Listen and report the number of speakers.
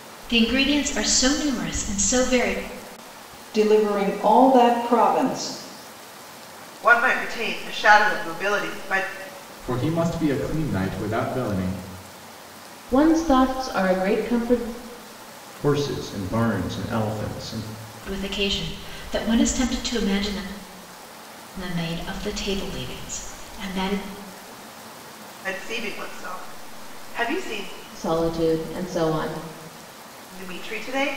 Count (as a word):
six